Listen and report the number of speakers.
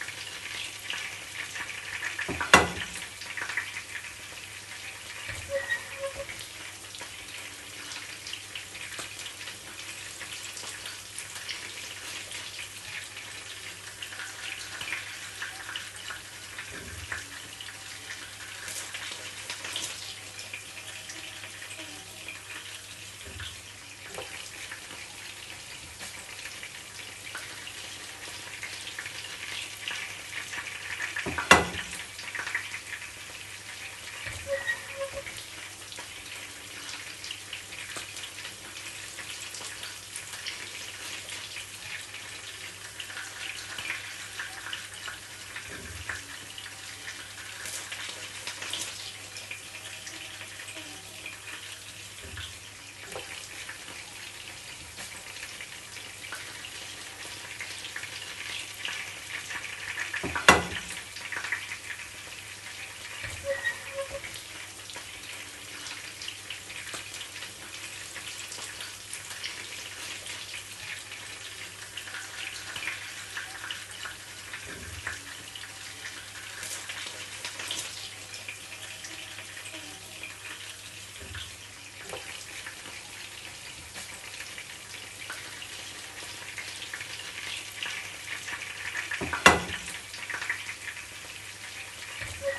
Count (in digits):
0